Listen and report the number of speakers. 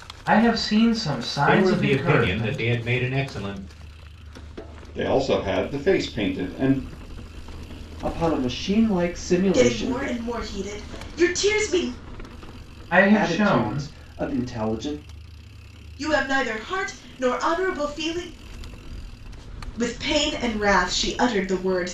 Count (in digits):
5